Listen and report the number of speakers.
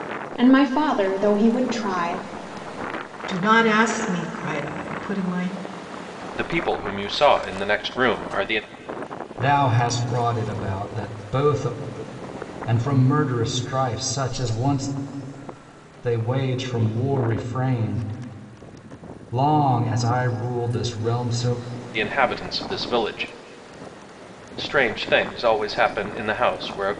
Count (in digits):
4